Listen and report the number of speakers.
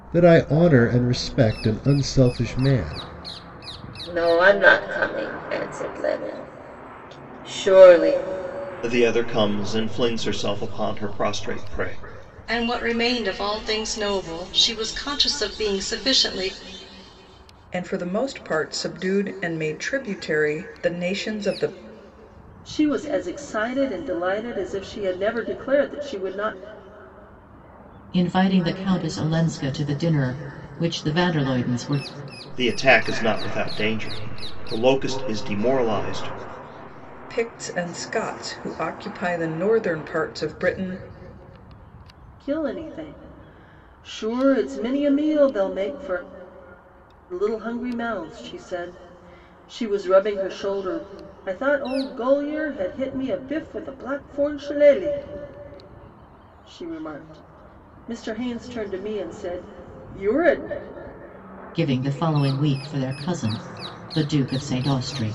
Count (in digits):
7